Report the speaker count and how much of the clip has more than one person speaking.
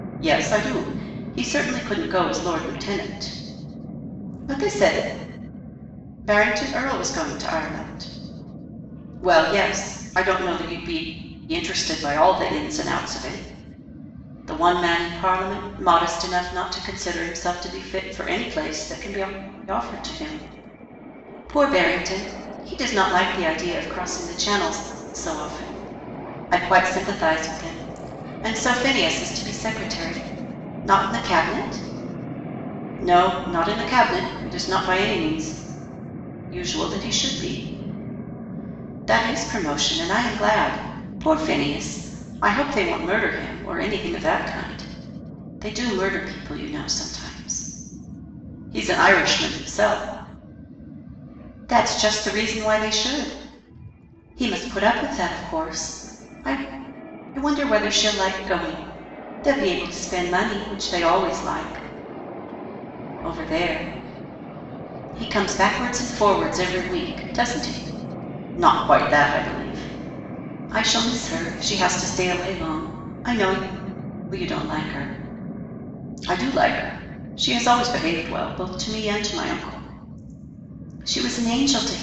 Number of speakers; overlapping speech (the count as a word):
one, no overlap